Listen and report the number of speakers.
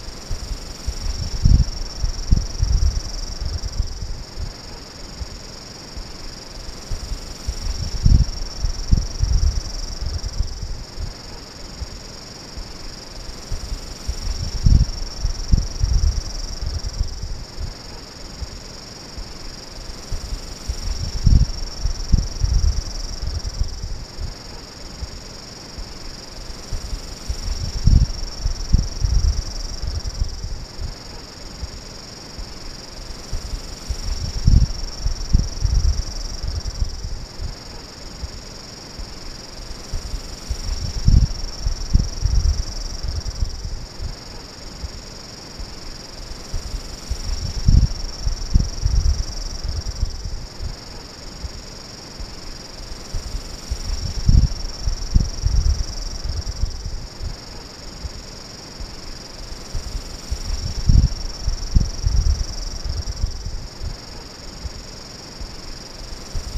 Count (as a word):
zero